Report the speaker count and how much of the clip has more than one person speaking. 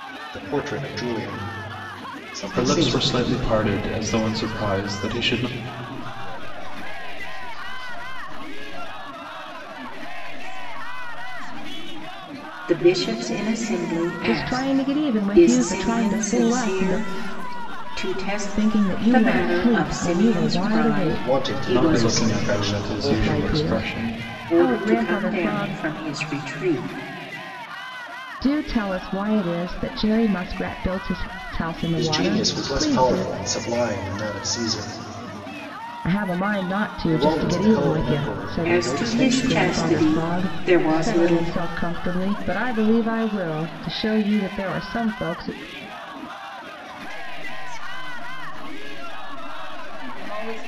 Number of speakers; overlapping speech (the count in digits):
6, about 38%